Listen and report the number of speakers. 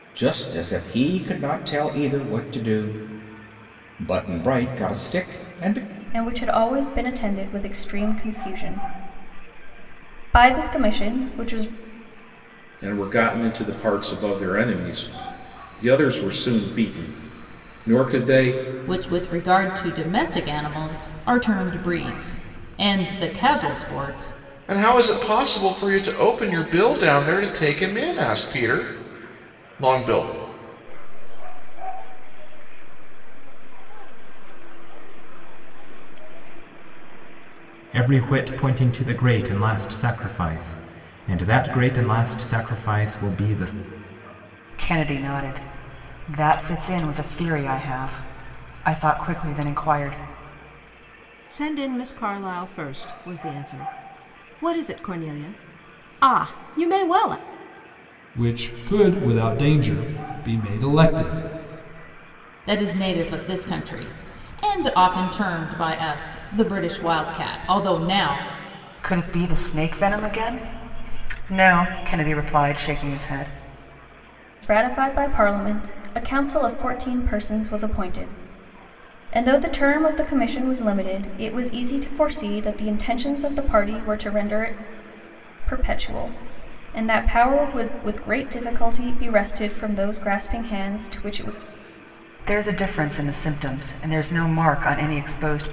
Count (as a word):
ten